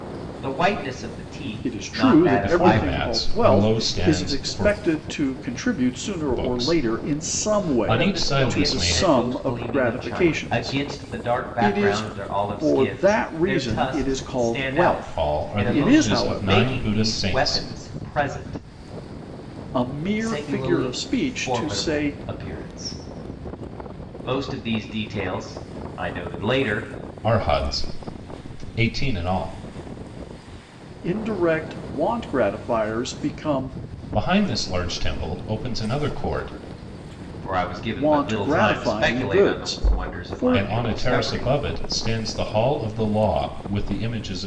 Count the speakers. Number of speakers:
three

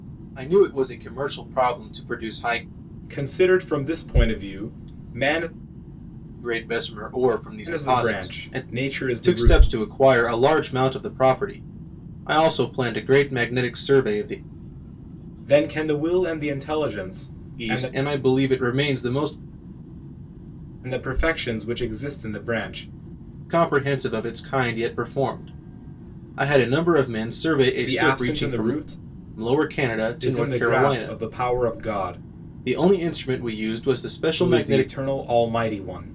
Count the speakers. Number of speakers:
two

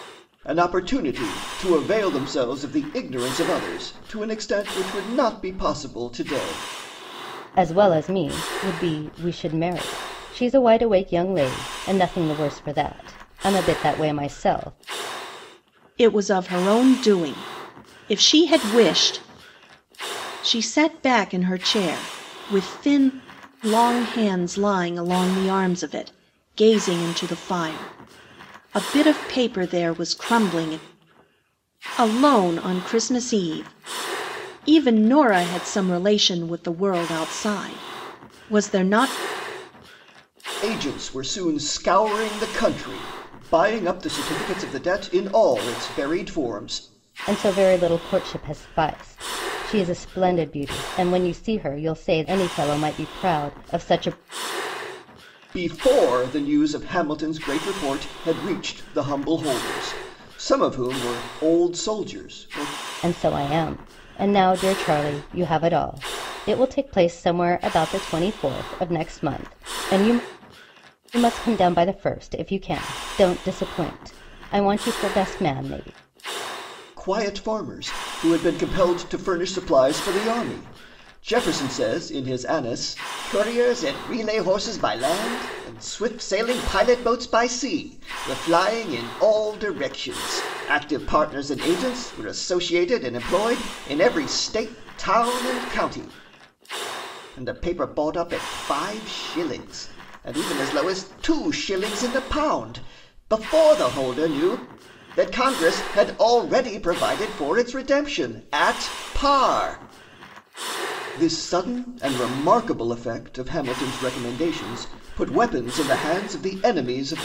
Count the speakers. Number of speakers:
three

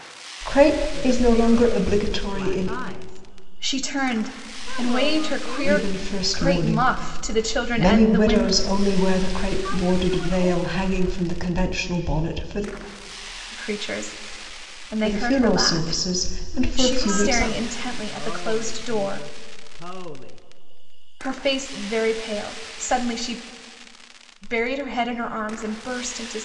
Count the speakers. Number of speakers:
three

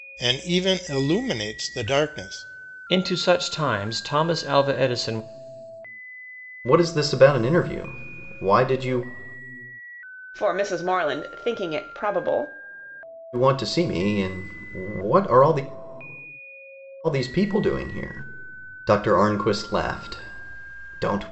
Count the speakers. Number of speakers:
four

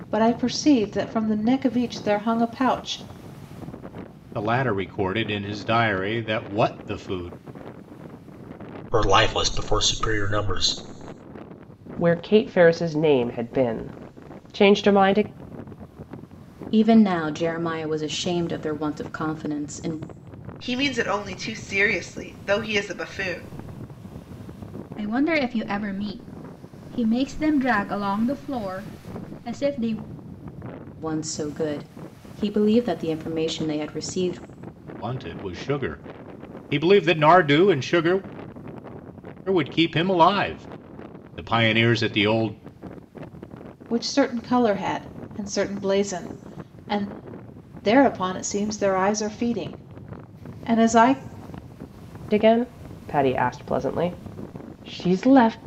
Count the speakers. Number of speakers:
seven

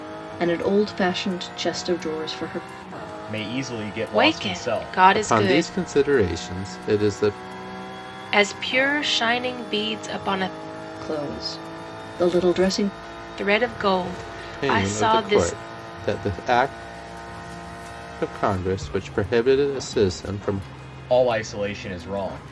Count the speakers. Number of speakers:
four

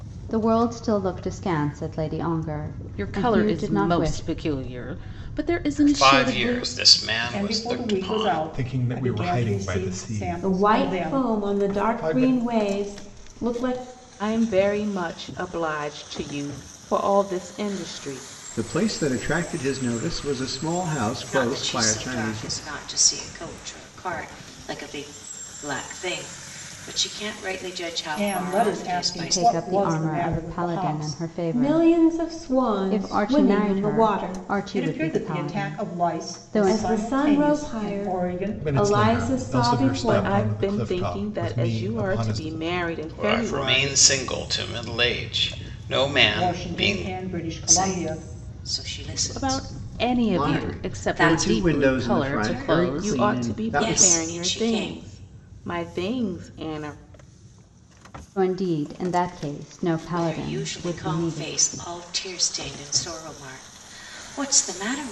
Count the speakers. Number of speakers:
nine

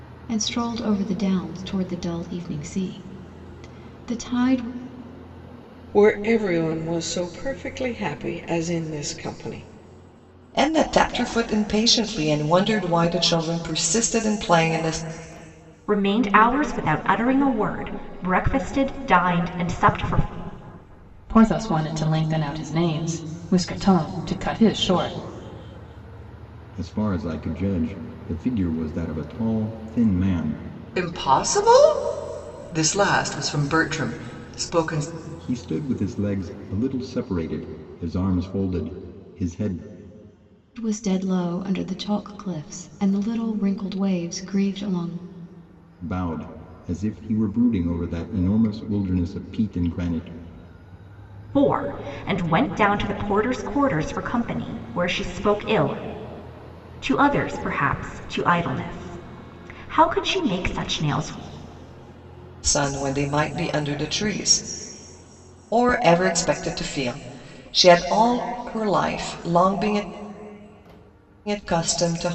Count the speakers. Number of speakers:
seven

